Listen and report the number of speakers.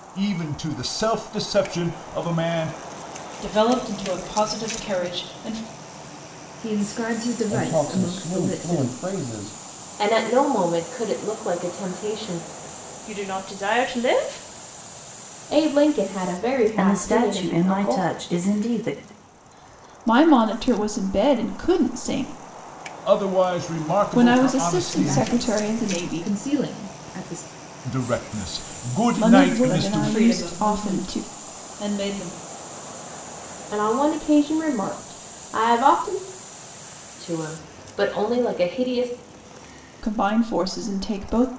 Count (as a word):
nine